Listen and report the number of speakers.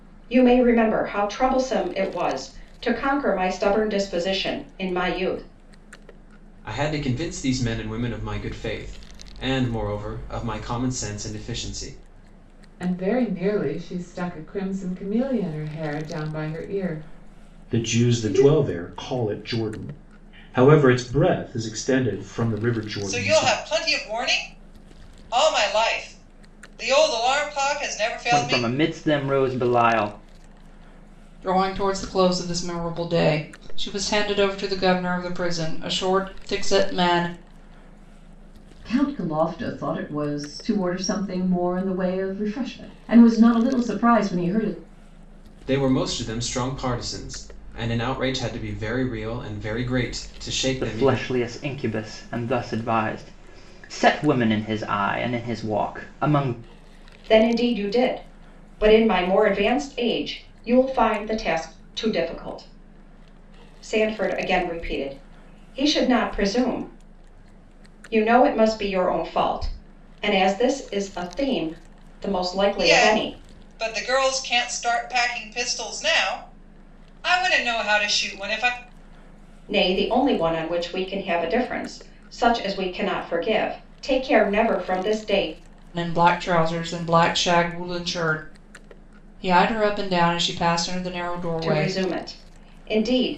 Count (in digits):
8